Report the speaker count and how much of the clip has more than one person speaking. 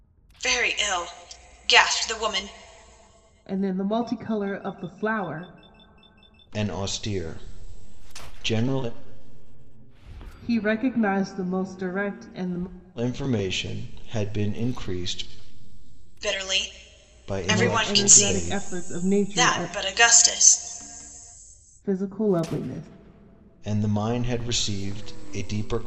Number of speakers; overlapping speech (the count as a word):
three, about 8%